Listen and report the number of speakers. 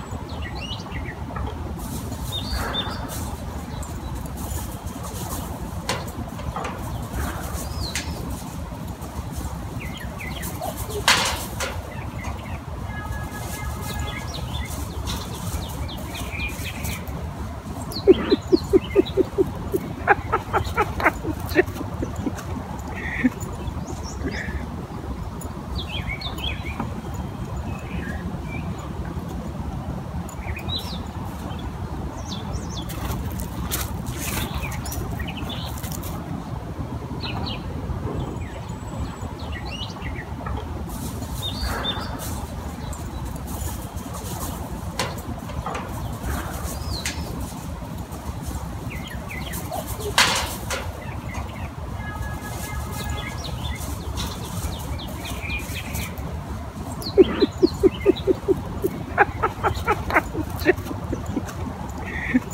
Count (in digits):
0